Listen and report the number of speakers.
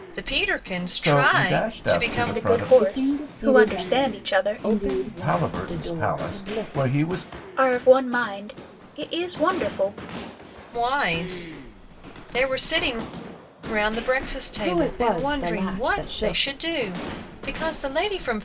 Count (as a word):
five